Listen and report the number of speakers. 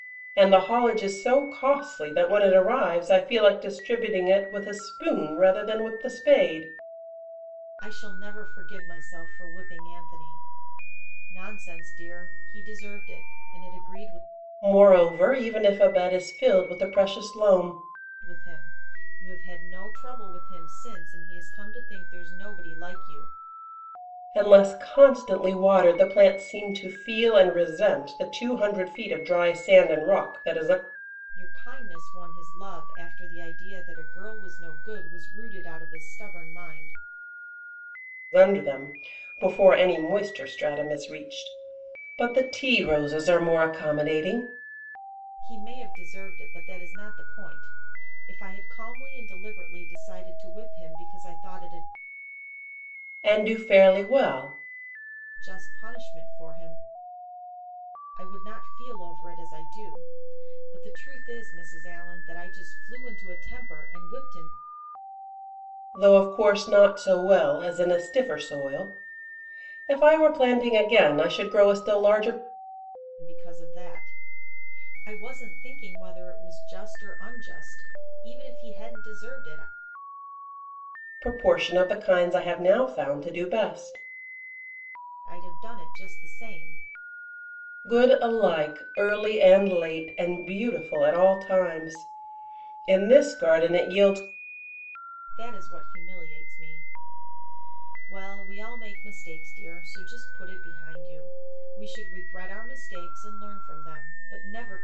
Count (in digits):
2